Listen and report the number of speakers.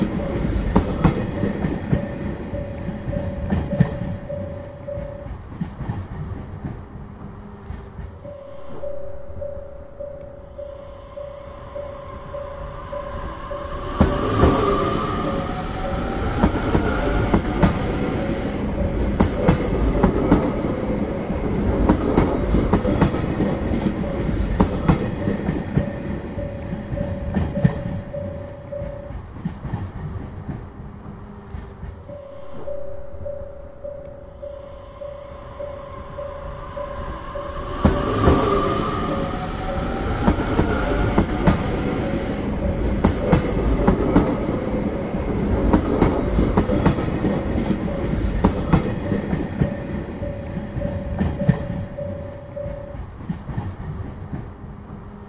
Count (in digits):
0